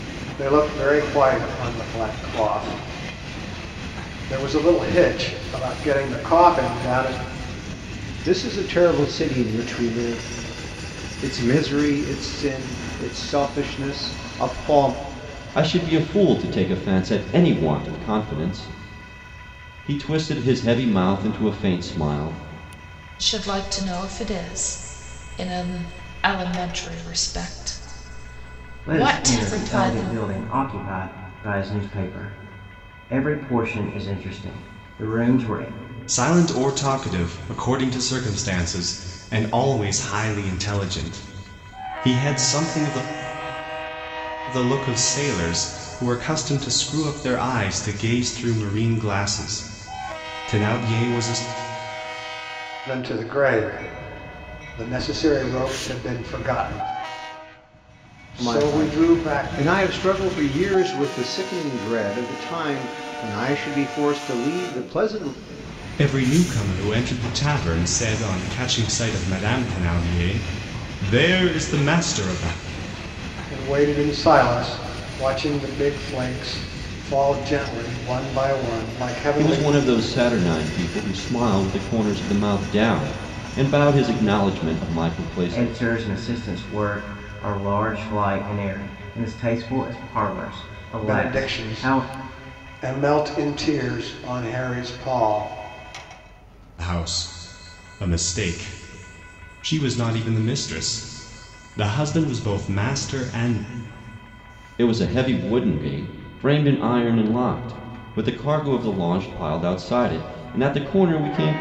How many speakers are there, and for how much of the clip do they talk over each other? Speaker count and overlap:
6, about 4%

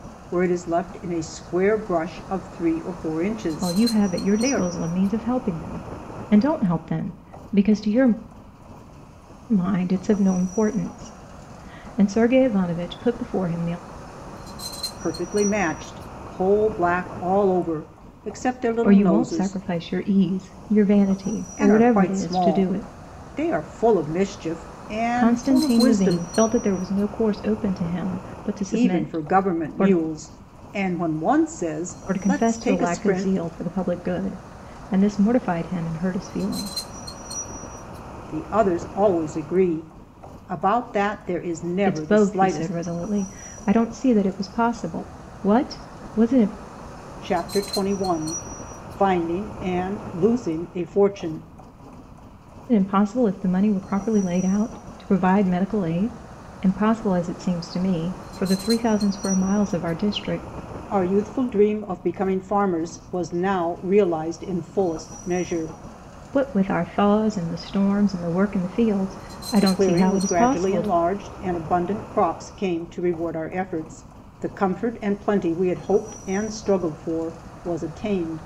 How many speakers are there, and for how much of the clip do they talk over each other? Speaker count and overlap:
2, about 12%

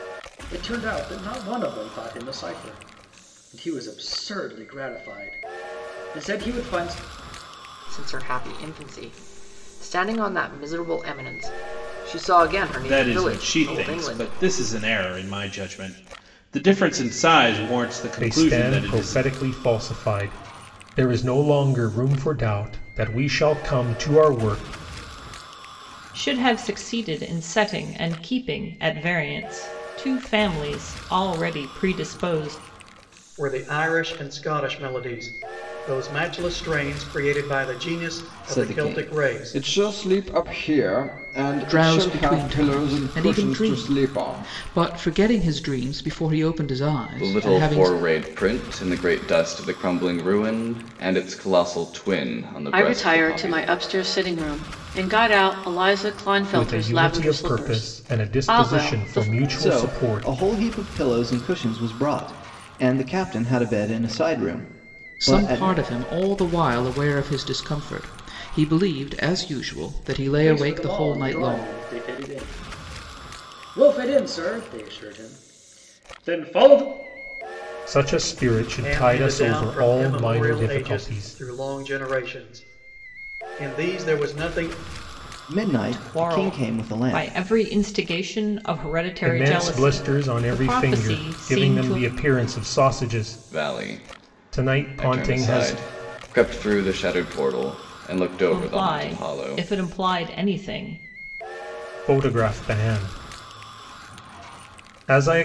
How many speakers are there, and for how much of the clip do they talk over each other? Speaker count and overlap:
10, about 23%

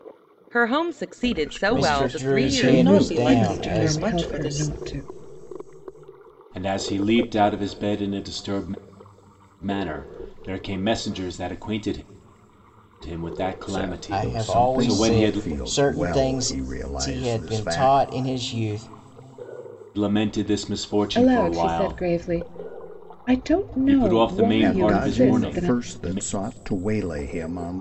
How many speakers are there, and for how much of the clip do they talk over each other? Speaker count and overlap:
6, about 39%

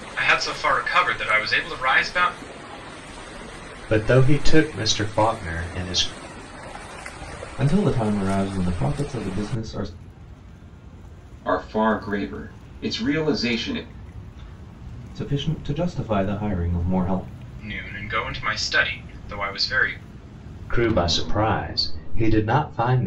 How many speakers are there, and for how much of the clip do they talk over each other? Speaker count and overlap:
4, no overlap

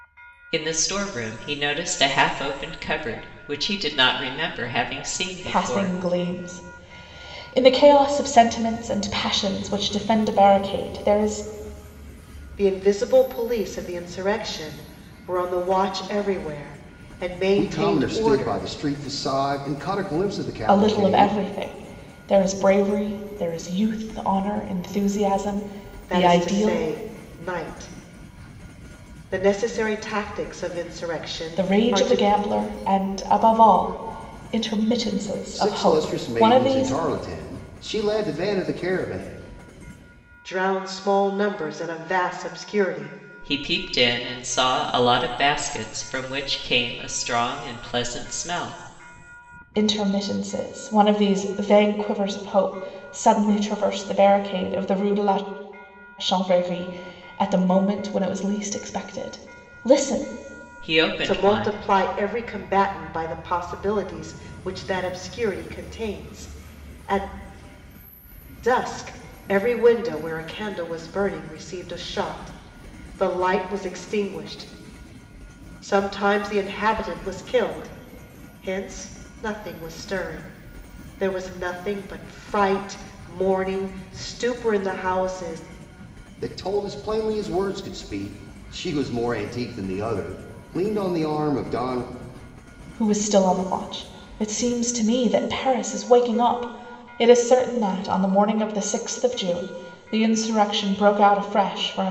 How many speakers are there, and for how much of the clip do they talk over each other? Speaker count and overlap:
4, about 6%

